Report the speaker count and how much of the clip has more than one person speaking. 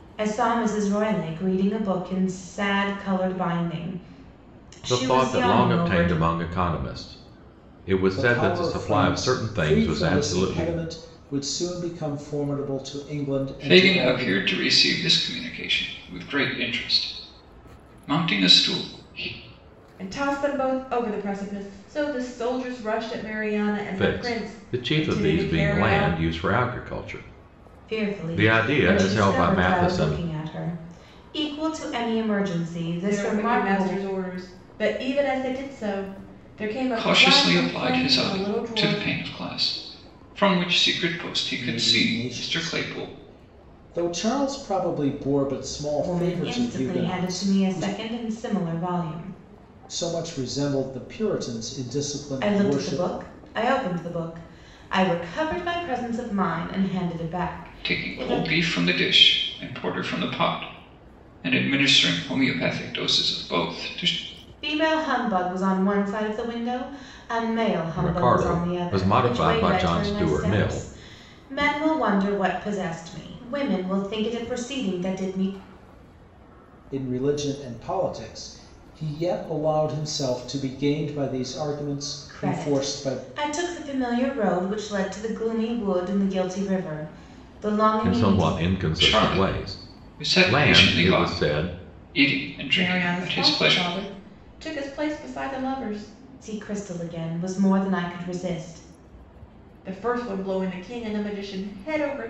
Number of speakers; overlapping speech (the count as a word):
five, about 25%